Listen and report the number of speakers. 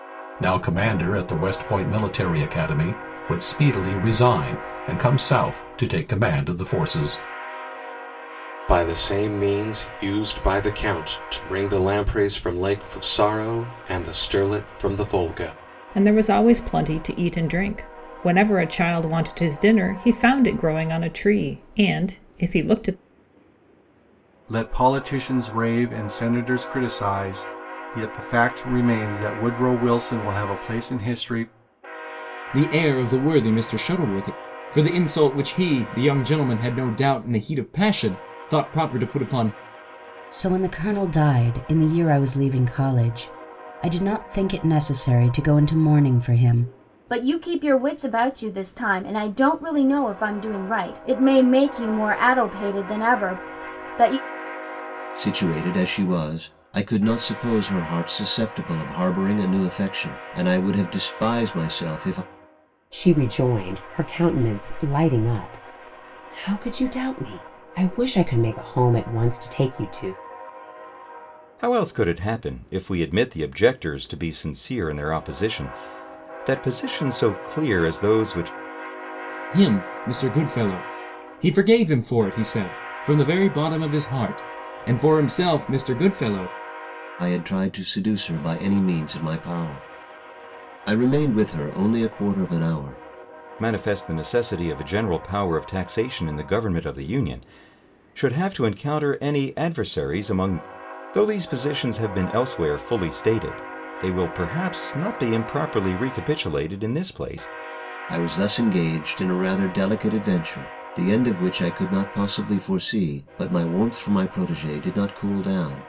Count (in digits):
10